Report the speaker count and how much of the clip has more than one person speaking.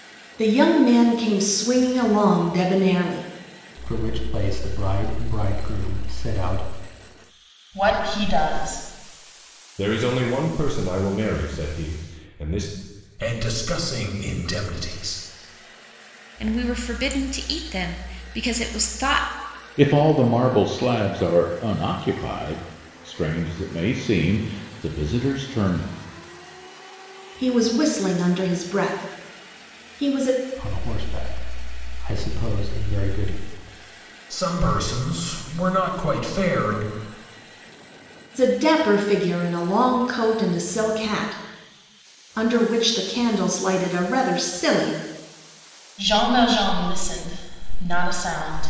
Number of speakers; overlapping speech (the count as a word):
seven, no overlap